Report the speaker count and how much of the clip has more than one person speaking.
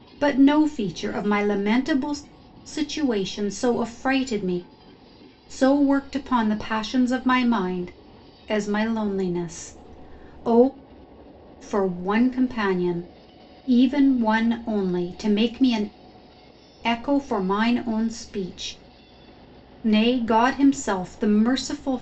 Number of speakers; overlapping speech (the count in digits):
1, no overlap